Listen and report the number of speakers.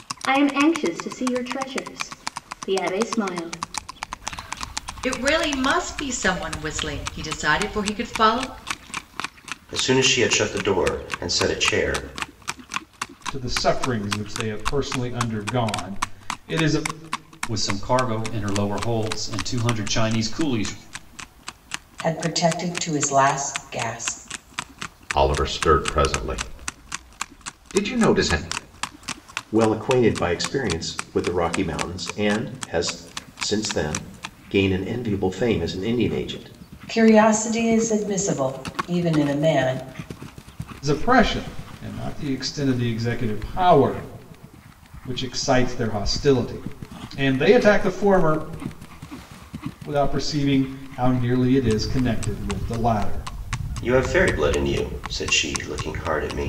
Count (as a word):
eight